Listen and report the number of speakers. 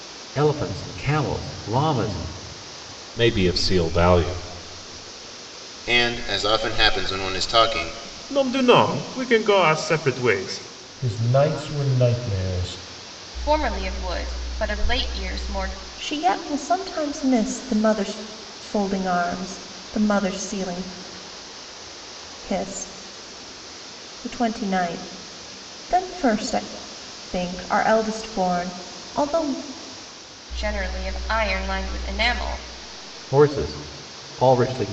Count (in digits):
7